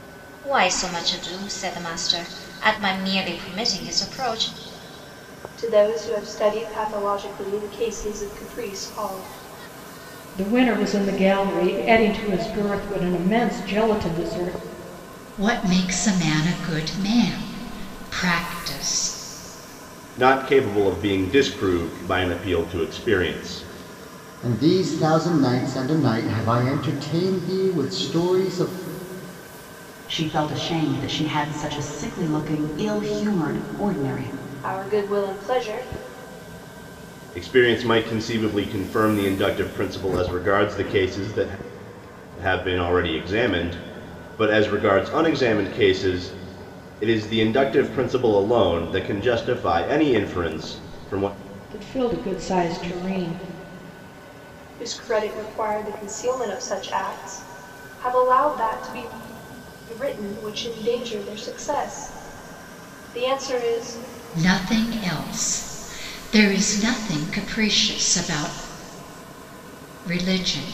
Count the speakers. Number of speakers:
7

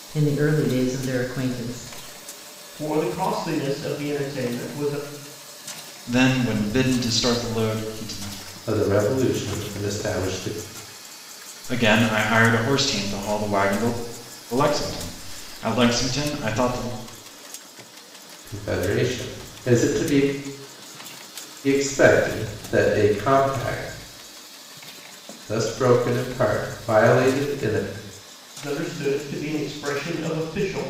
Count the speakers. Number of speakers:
4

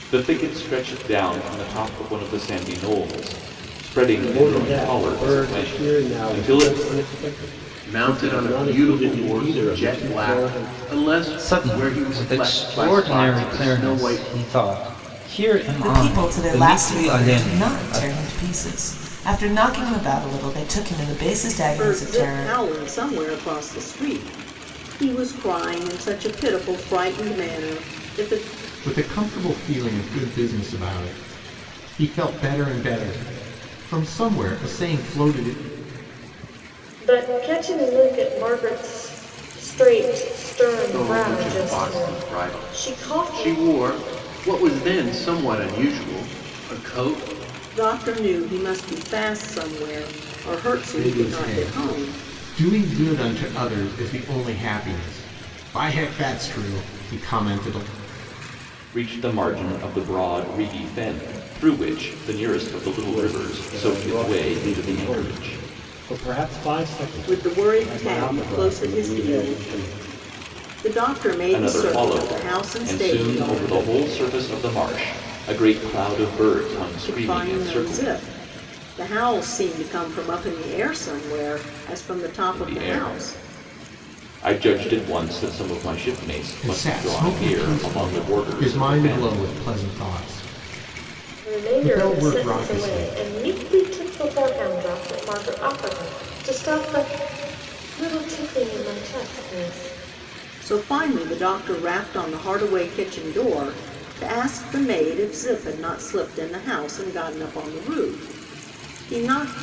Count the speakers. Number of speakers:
8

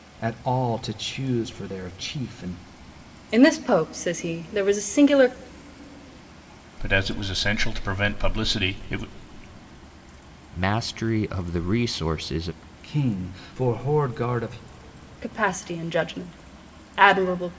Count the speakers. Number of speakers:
4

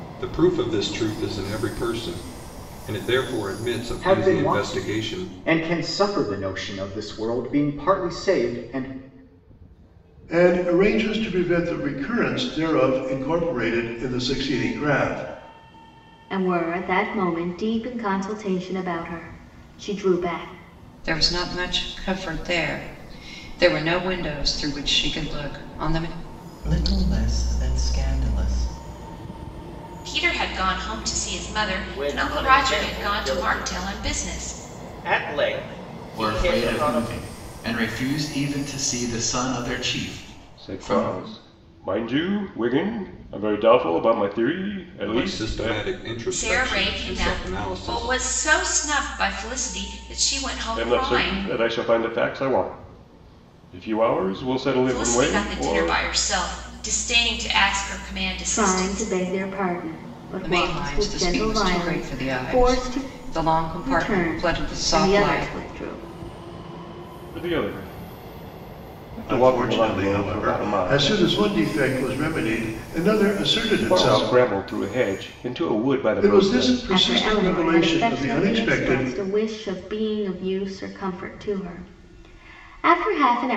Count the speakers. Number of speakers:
10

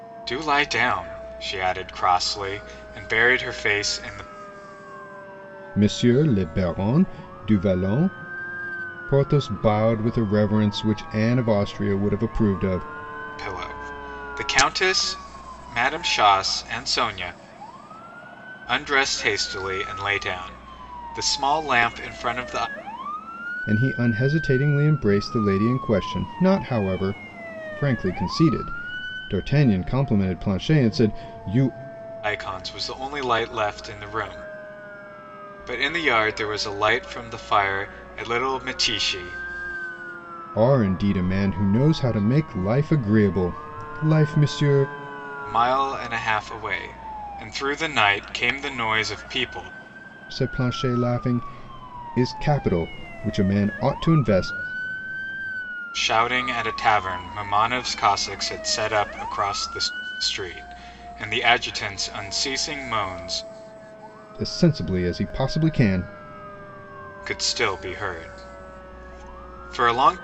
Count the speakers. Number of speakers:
2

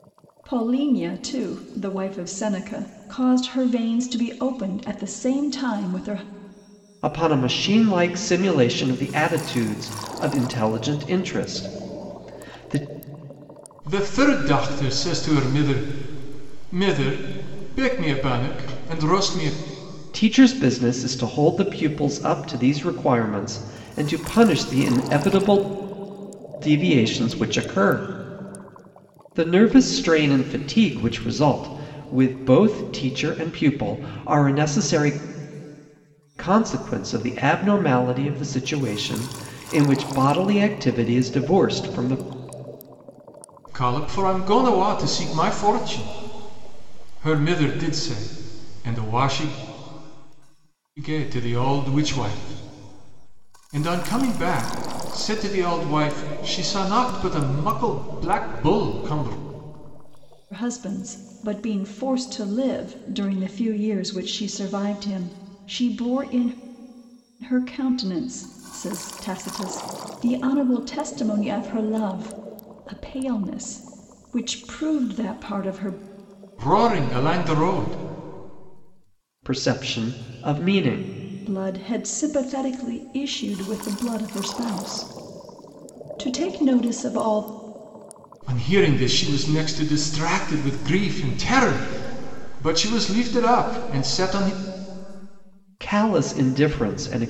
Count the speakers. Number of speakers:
3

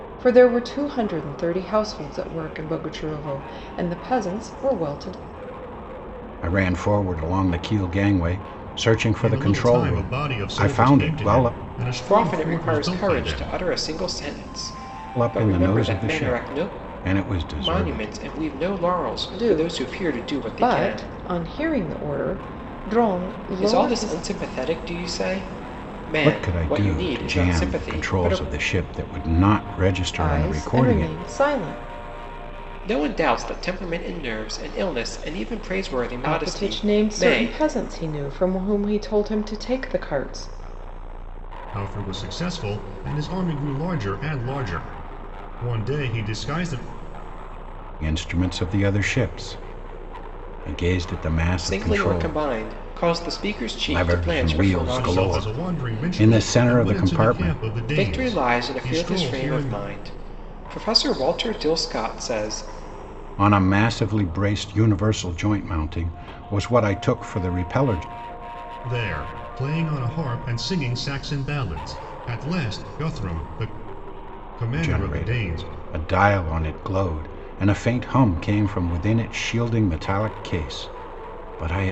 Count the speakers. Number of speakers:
4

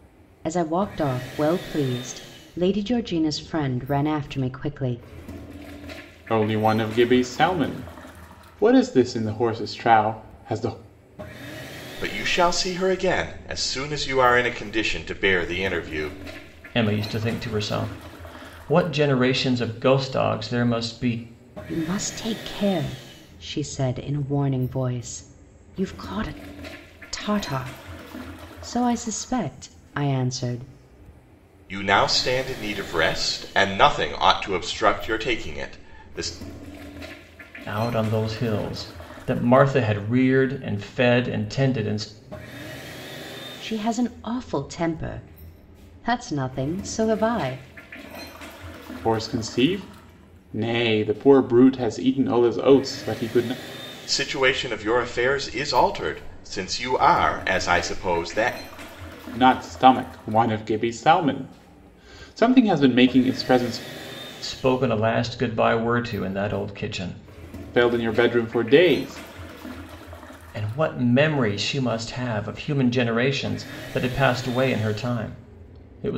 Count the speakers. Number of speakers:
4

